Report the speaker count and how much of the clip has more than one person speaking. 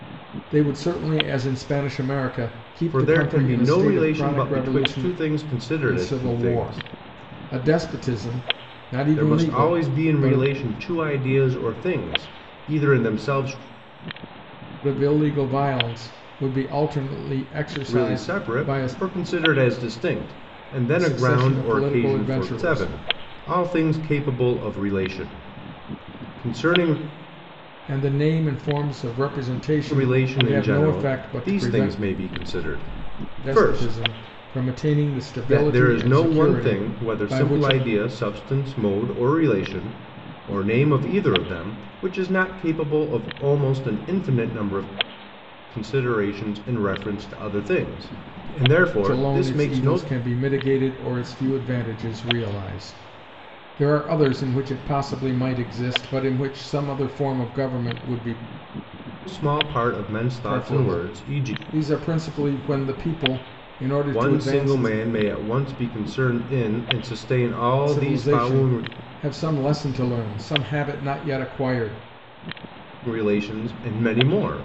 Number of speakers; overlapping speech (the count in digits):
2, about 22%